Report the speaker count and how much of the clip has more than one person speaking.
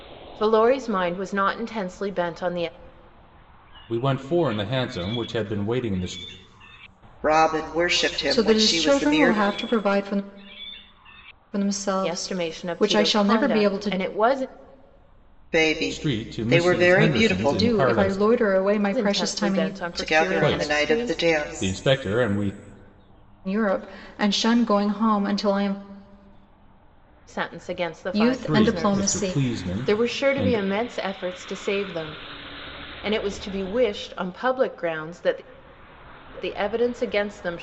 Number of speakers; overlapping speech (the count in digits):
4, about 27%